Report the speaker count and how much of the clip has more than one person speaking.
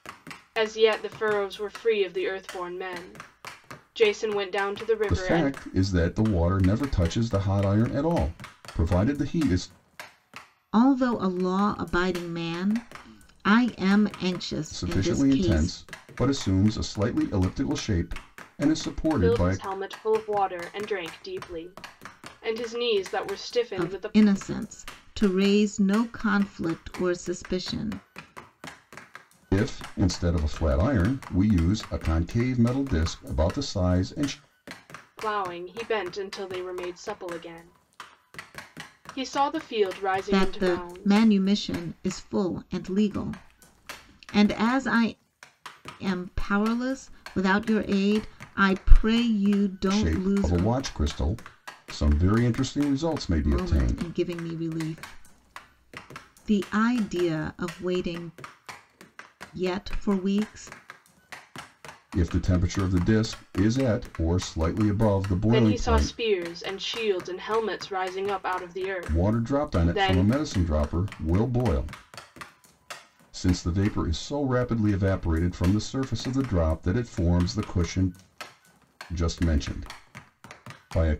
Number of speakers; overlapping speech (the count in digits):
3, about 9%